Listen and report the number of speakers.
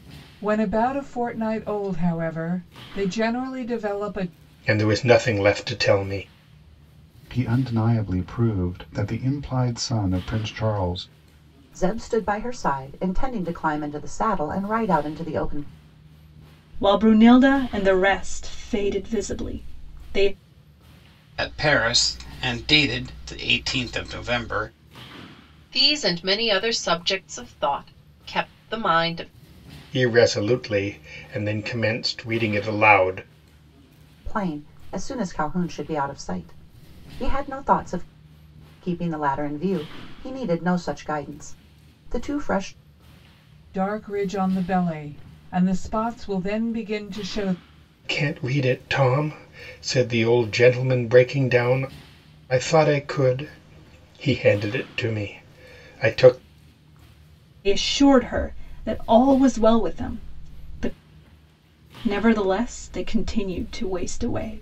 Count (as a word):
seven